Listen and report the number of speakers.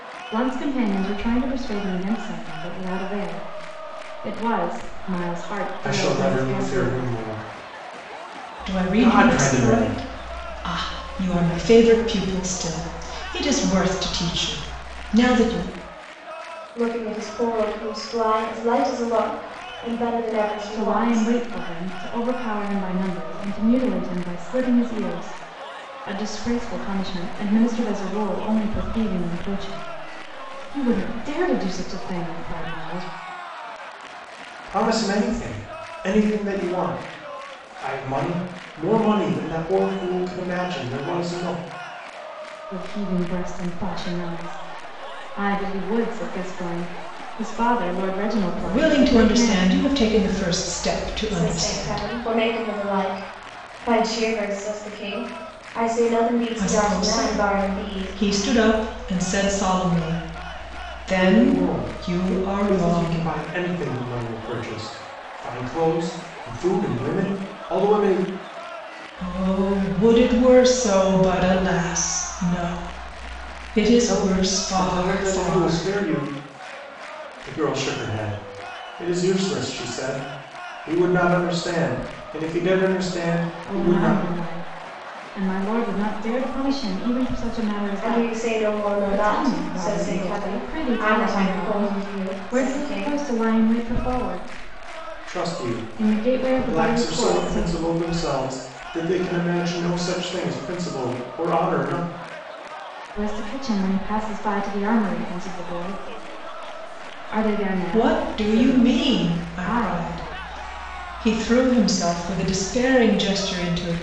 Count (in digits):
4